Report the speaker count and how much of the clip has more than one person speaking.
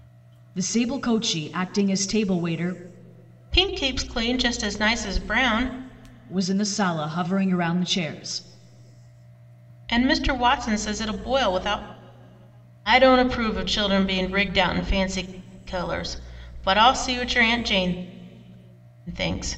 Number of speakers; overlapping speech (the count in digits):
2, no overlap